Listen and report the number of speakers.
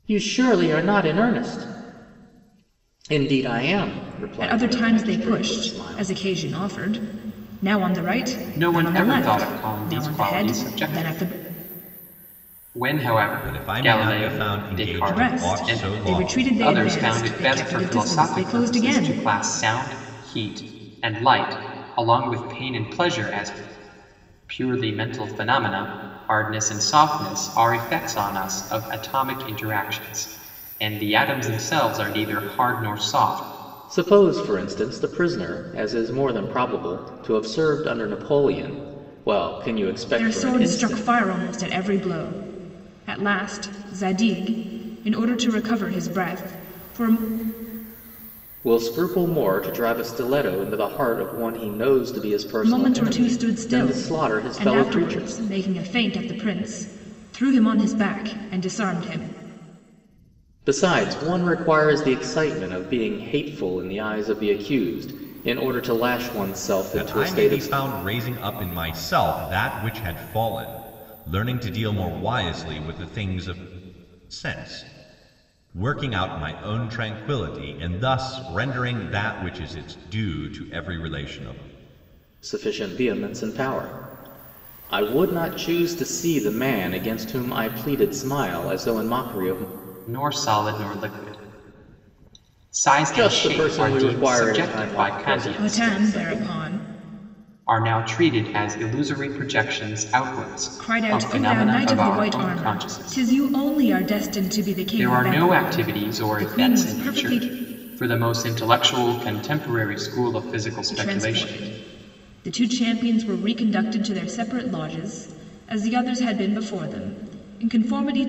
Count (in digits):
4